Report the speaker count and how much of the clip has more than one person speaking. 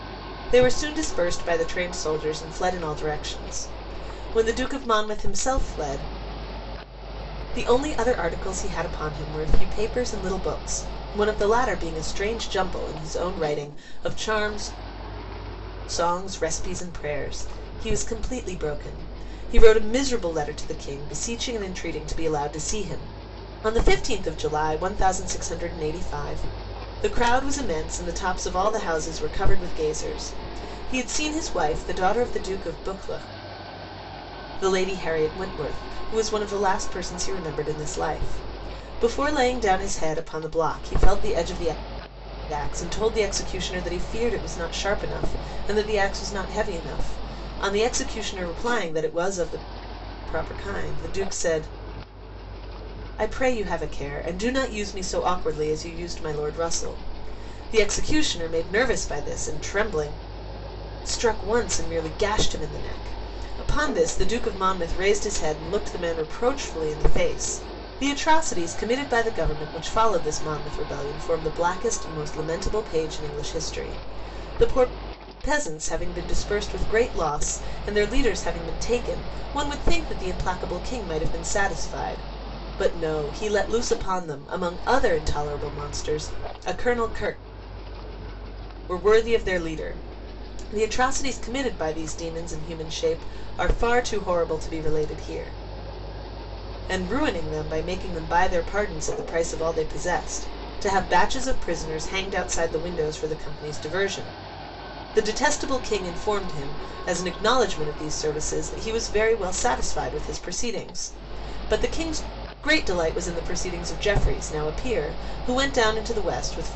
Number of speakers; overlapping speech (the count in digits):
1, no overlap